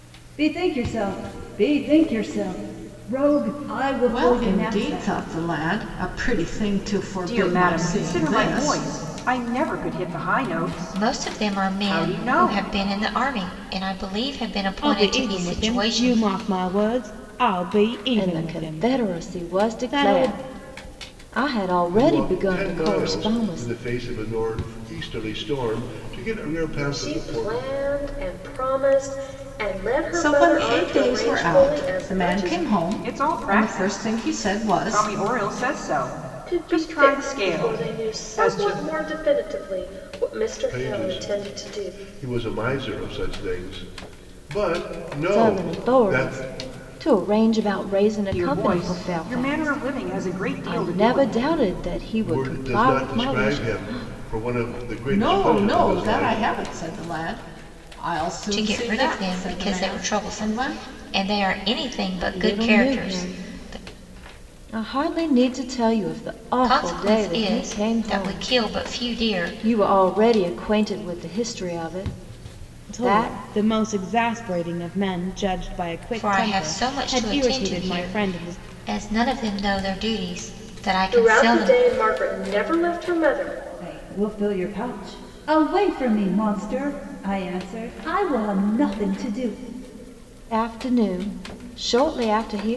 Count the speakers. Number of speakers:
8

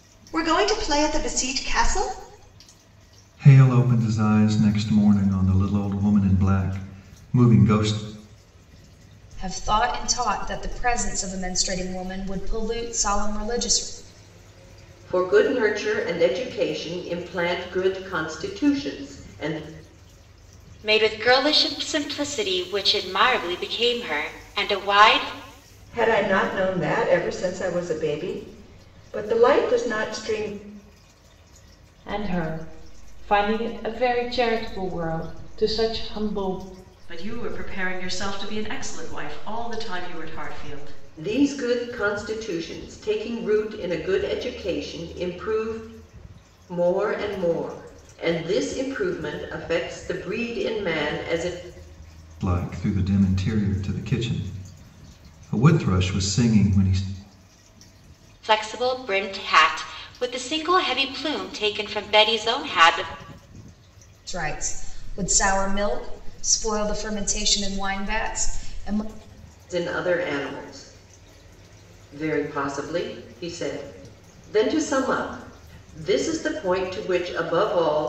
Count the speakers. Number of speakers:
8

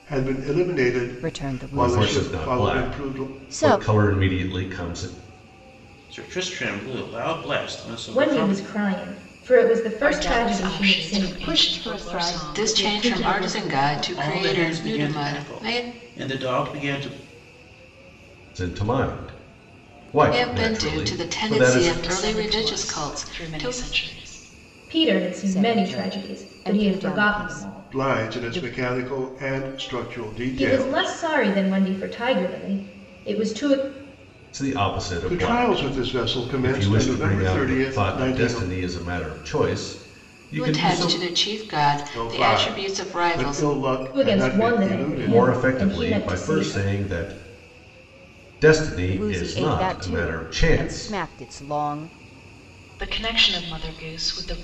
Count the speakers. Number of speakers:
8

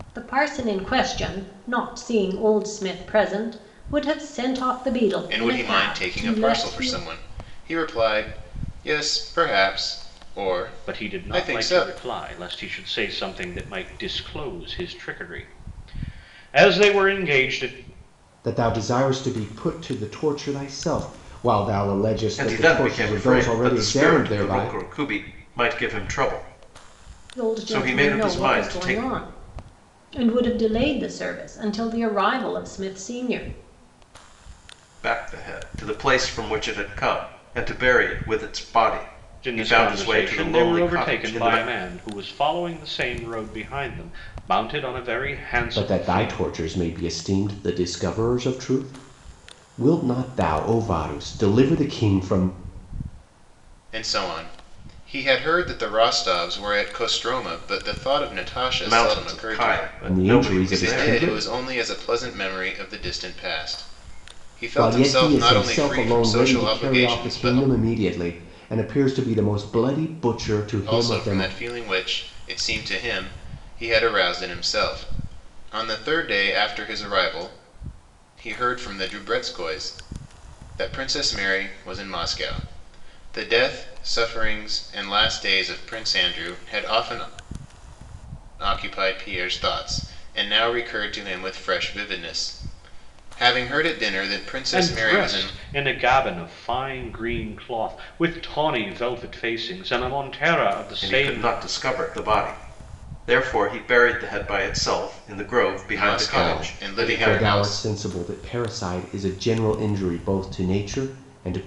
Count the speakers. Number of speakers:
5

